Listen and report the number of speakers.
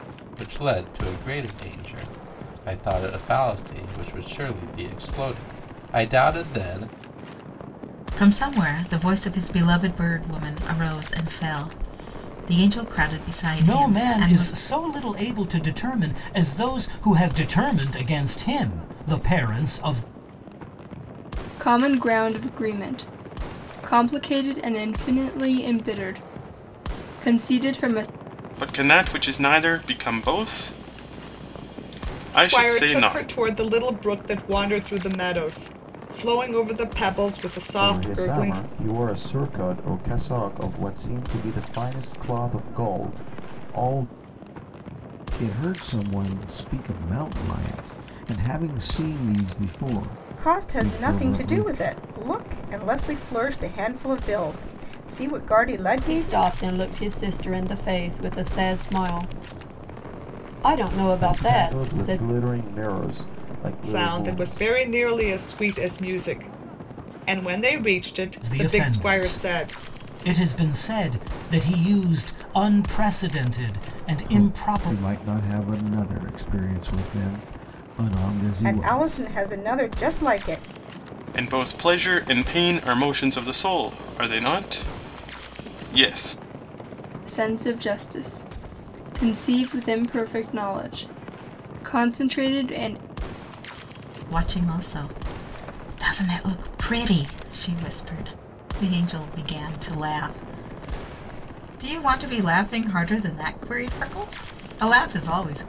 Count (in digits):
10